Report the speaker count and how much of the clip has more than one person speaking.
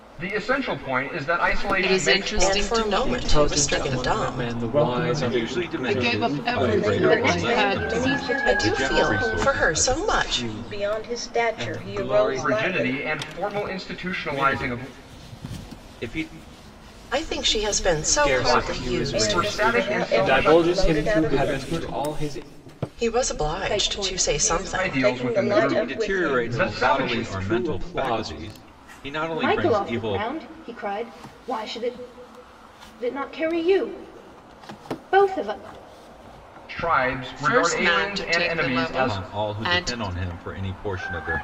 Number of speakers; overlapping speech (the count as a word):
ten, about 59%